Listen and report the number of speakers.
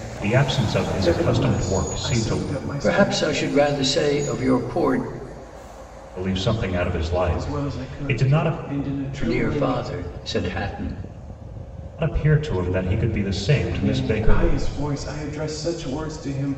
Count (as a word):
three